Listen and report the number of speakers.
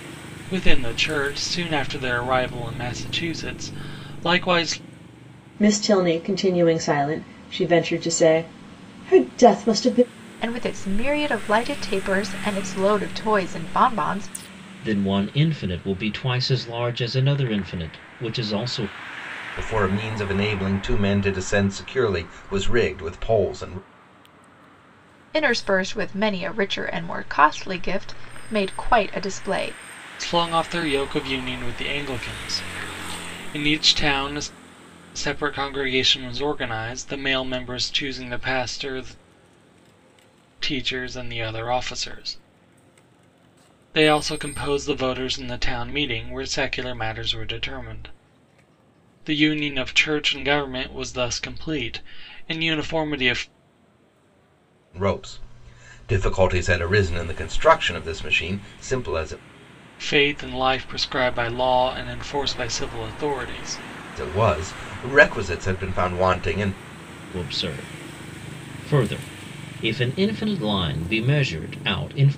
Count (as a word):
five